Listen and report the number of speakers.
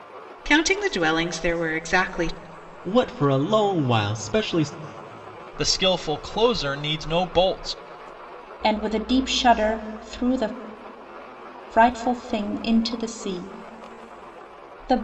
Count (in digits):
4